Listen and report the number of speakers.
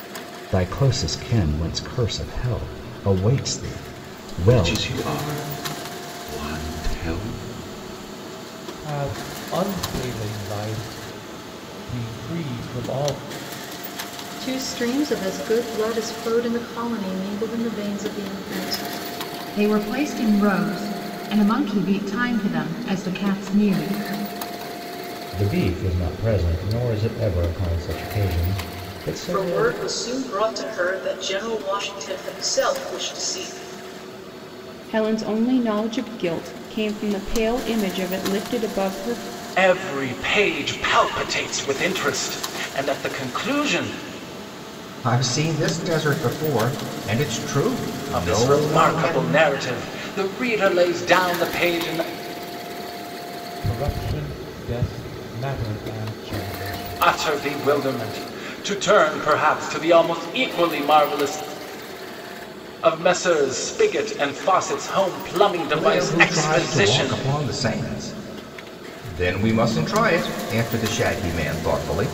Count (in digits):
10